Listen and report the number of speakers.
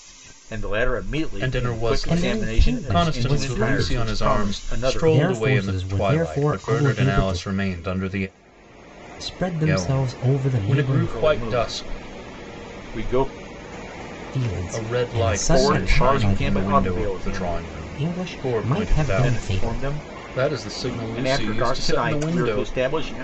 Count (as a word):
three